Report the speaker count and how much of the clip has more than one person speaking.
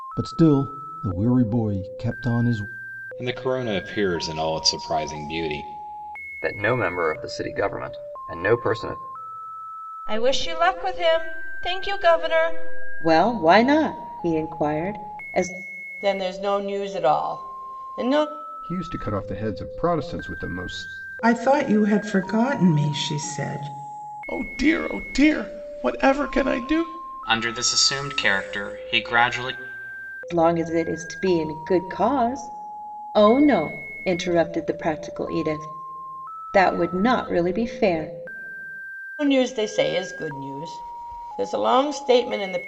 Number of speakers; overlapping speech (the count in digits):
10, no overlap